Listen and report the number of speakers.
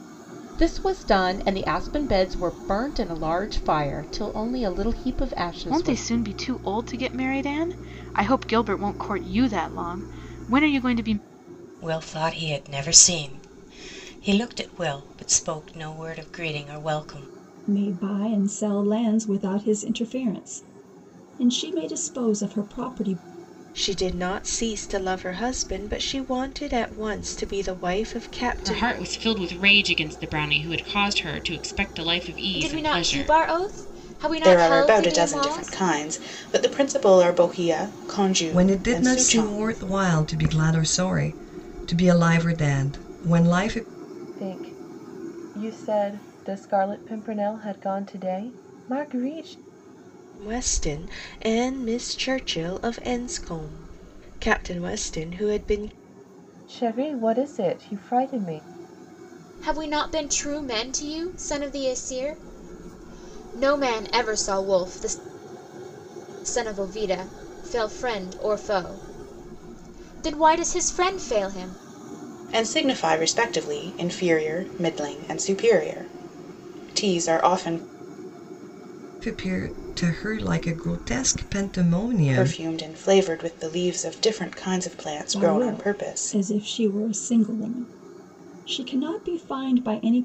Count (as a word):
ten